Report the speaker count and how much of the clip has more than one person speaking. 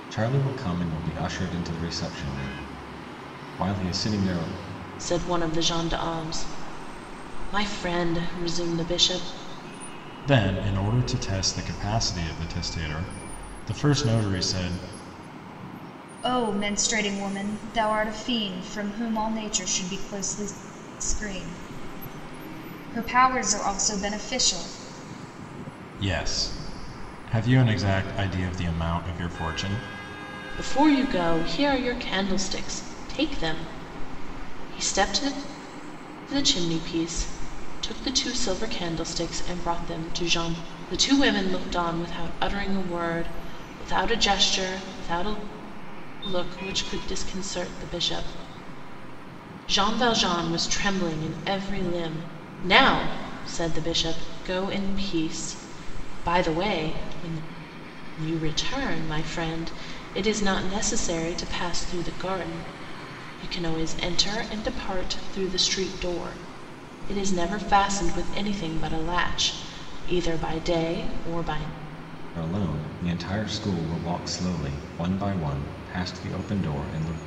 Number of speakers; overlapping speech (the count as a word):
four, no overlap